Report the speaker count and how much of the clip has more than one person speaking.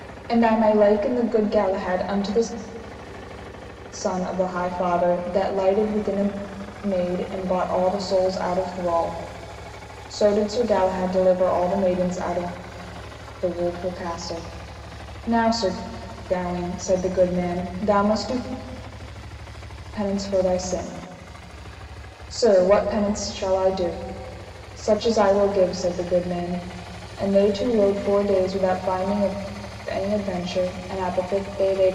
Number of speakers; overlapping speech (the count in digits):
1, no overlap